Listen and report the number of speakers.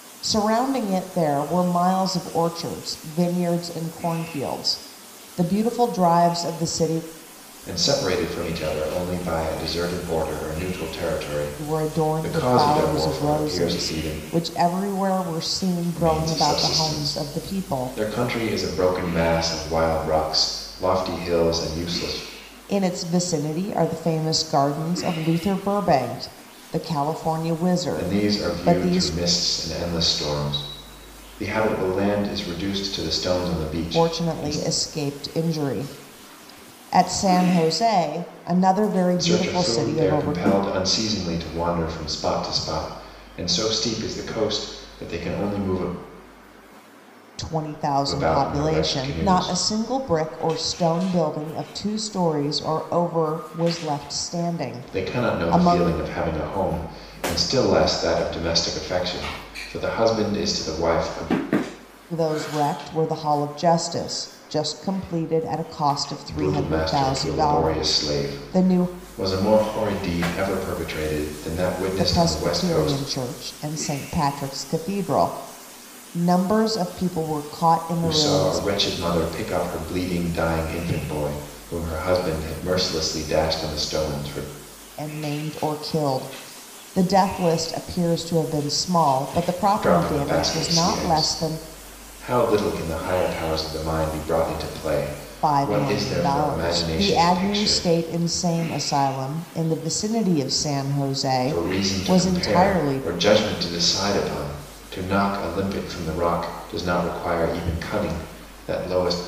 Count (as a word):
two